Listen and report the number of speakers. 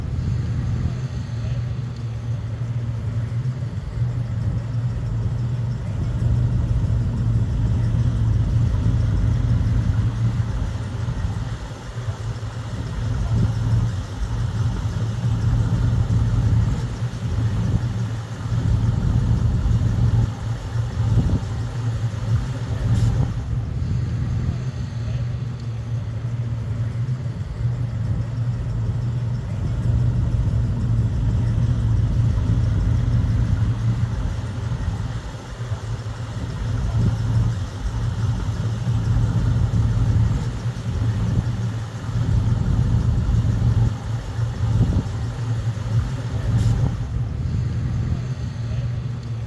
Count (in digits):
0